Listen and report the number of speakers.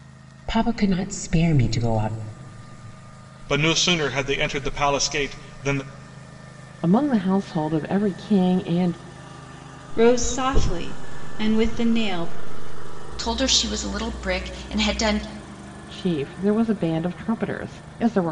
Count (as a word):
five